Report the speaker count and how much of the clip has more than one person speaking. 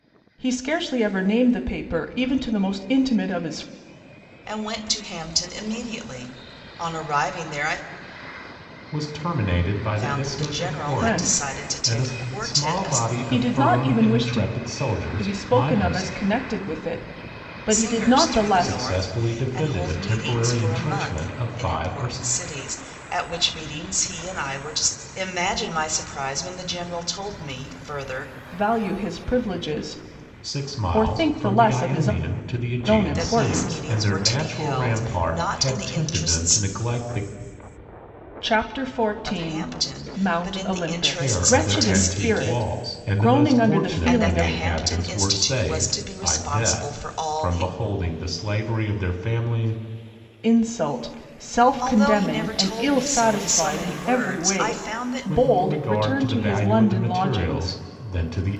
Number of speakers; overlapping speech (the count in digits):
3, about 51%